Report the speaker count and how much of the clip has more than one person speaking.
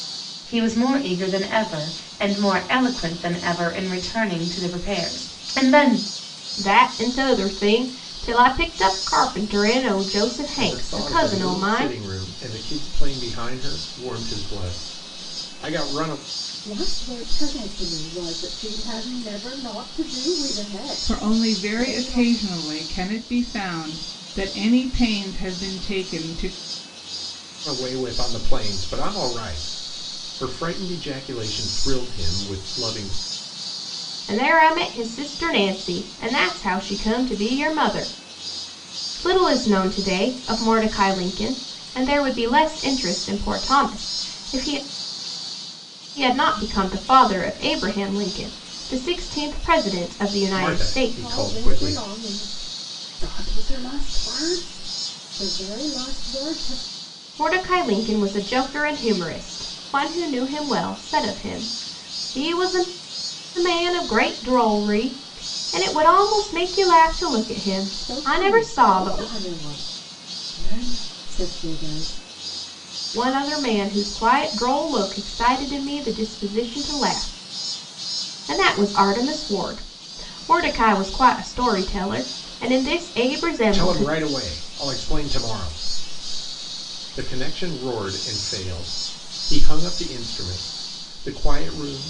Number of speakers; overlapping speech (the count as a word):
five, about 7%